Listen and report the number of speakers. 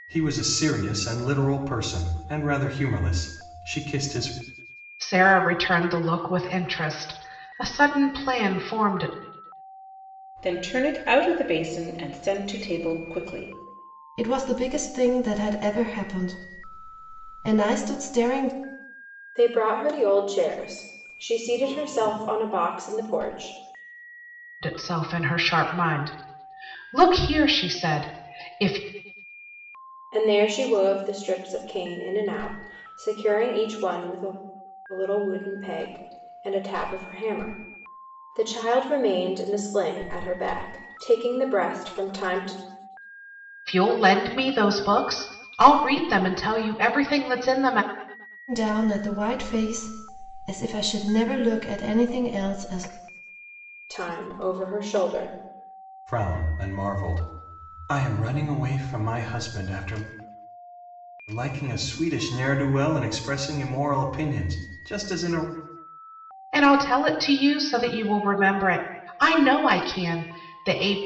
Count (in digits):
5